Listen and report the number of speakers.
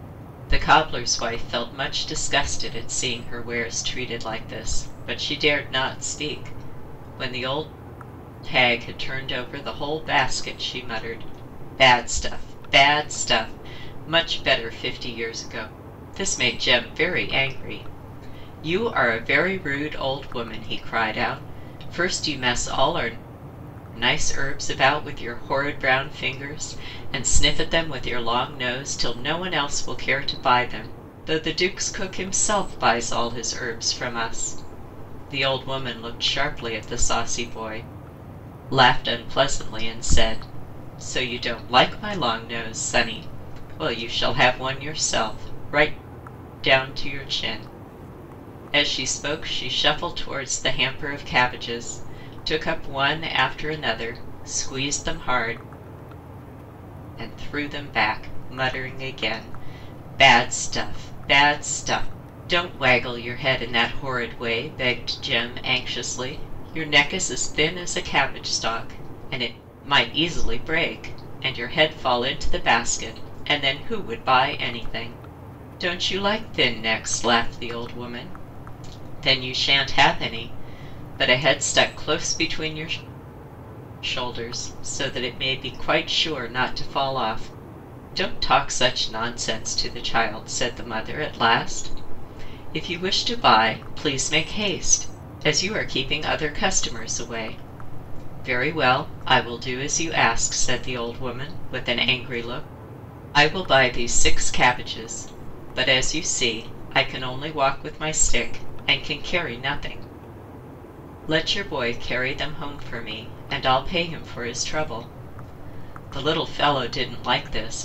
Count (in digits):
1